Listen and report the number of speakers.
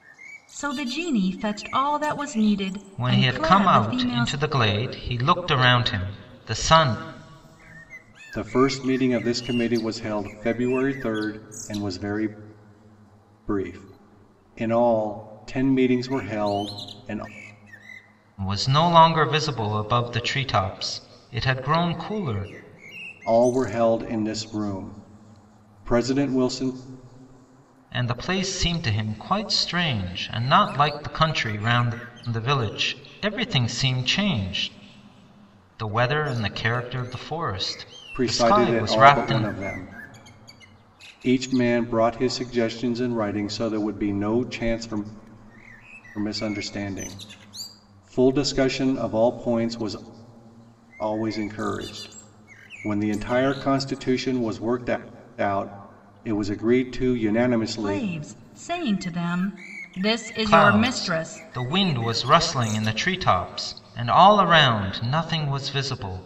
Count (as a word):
three